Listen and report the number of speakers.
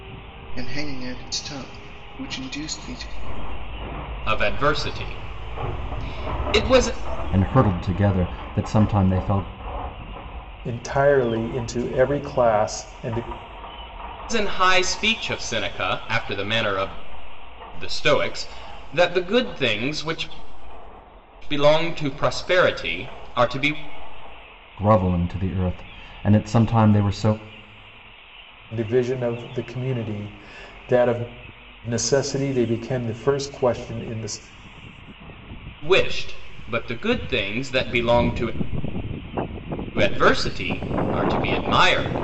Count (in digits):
4